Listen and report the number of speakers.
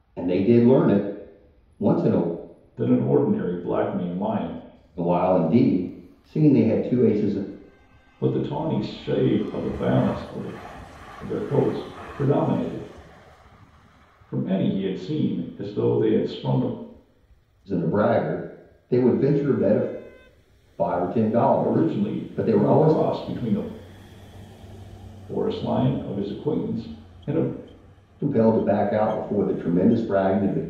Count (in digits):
2